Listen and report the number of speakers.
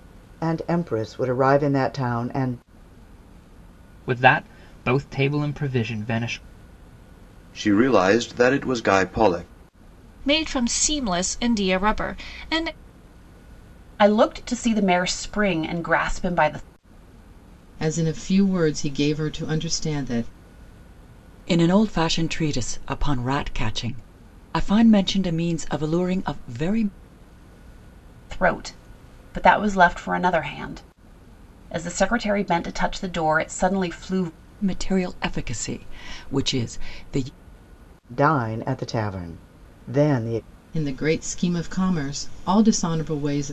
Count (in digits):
7